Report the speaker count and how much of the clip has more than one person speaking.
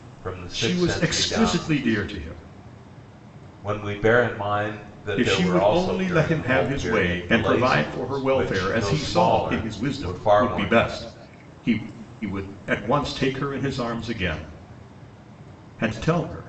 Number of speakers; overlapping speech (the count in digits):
2, about 43%